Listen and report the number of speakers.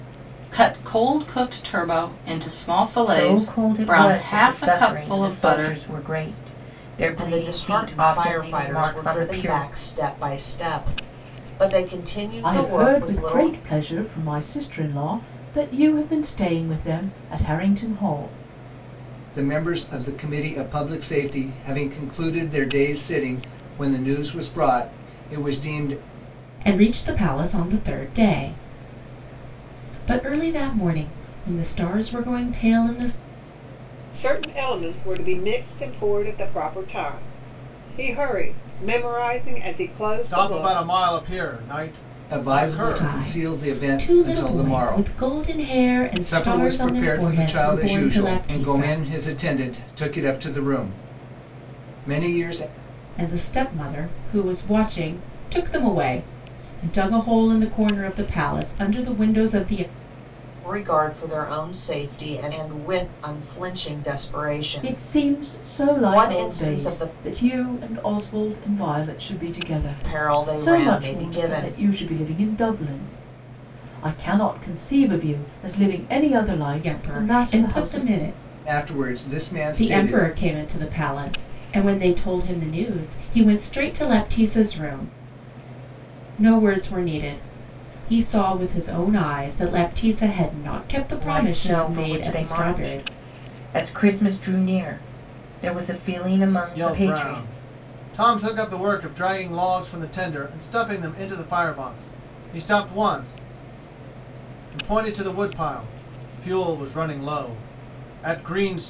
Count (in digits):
8